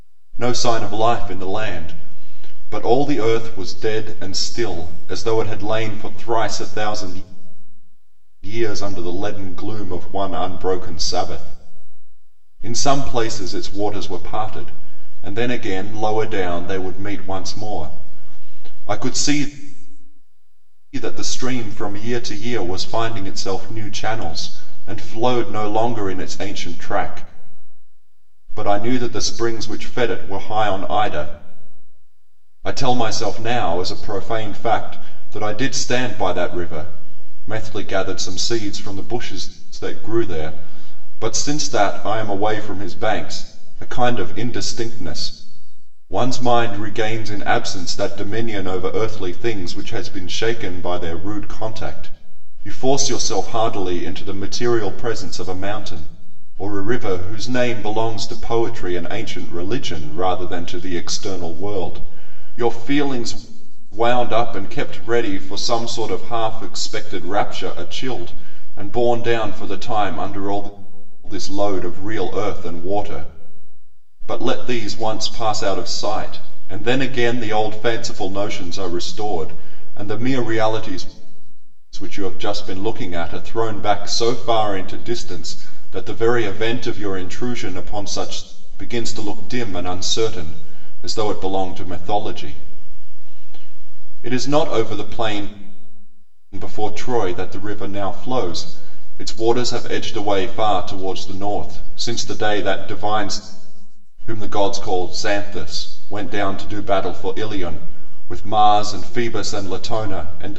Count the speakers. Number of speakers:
one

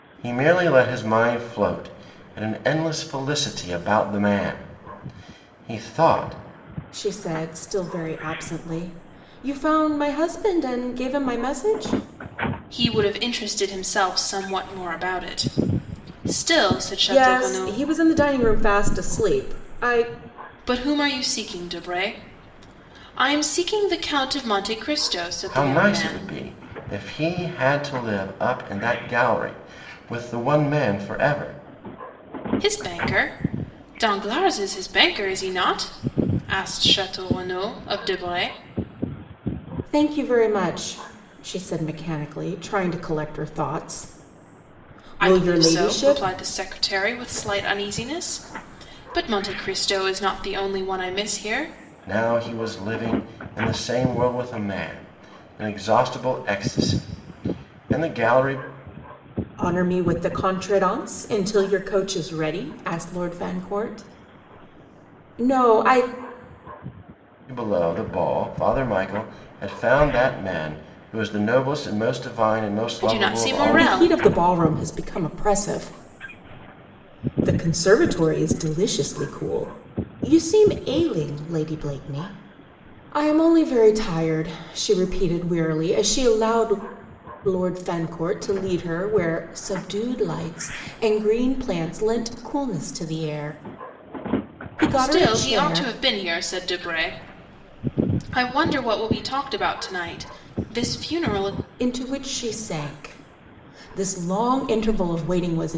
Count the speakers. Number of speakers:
three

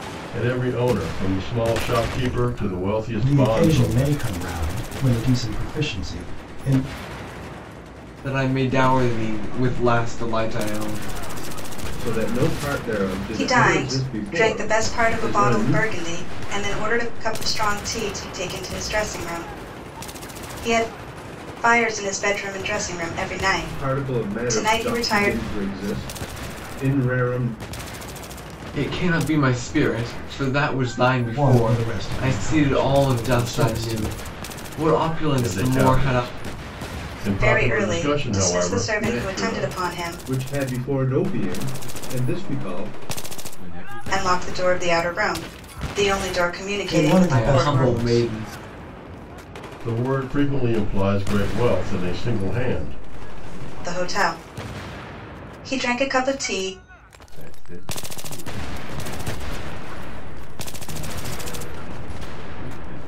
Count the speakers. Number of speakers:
six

